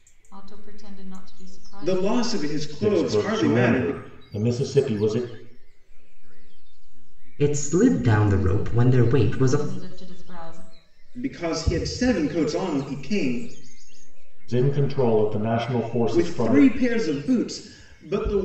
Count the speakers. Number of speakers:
5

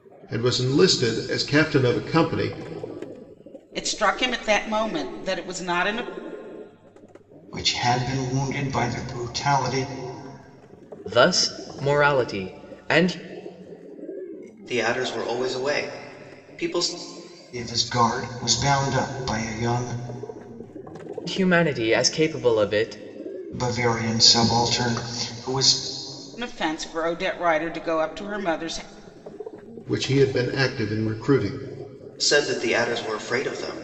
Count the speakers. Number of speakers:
5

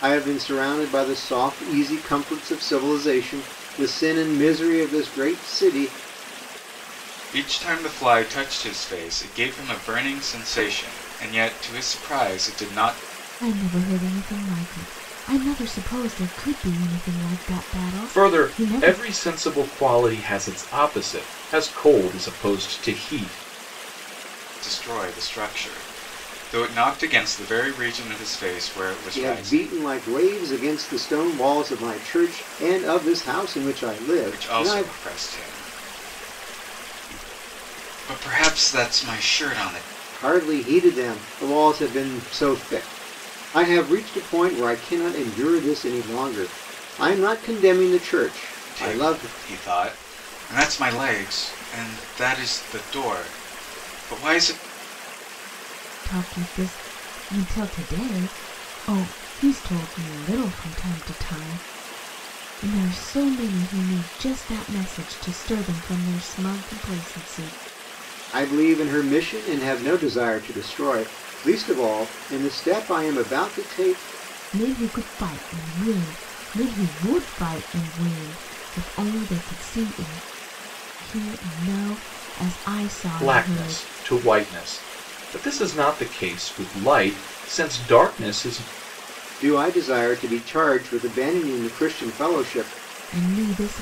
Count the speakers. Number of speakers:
4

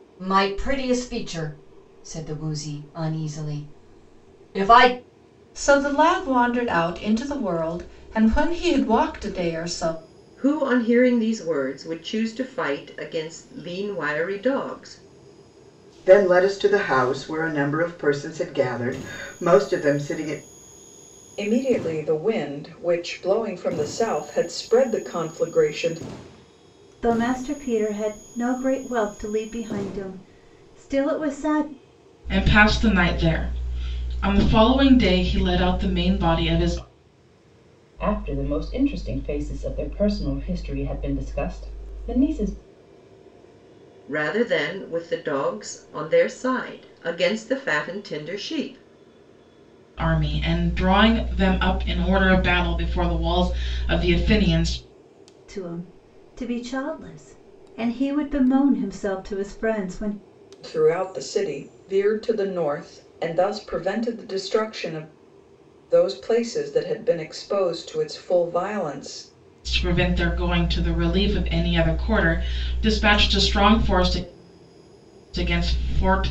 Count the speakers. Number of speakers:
8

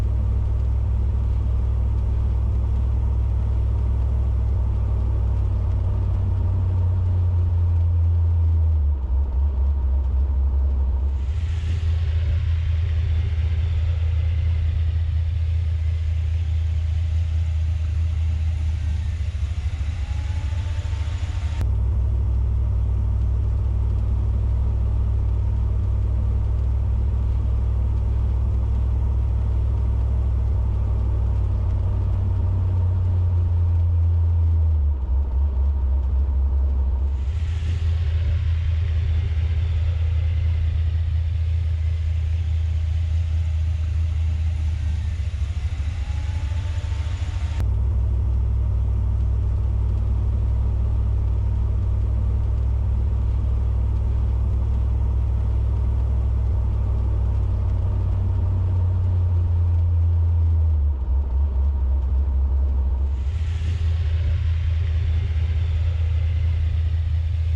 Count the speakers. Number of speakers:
0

